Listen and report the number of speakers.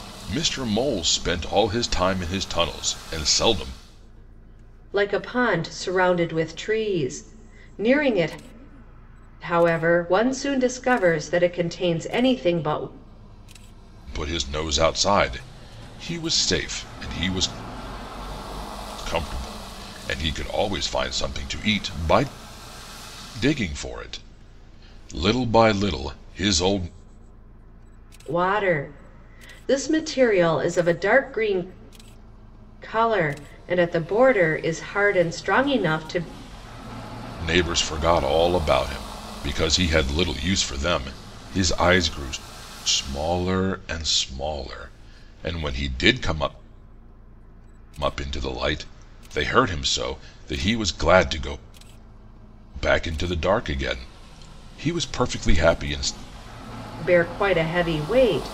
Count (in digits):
2